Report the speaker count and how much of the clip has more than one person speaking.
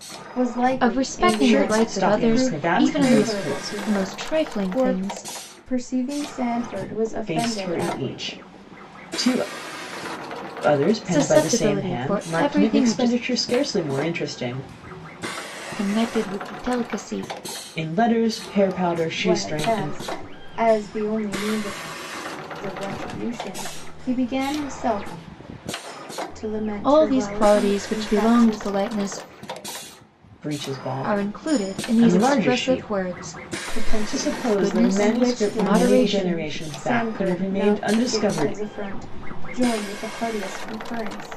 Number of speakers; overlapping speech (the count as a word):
three, about 40%